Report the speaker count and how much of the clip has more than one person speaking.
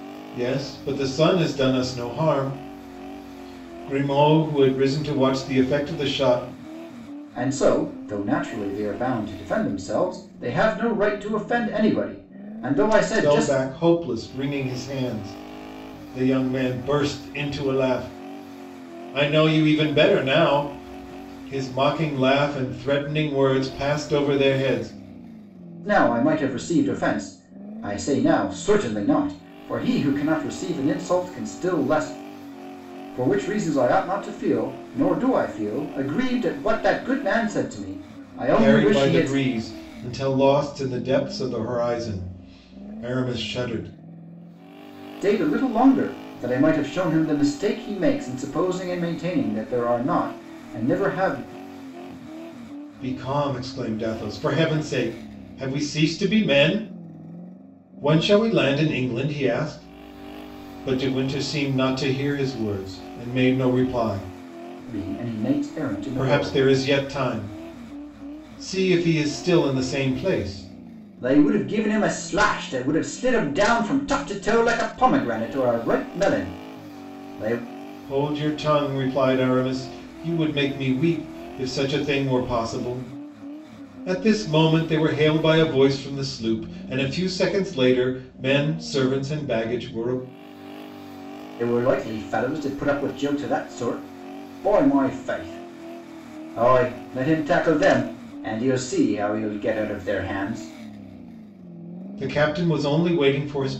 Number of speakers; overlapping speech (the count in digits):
2, about 2%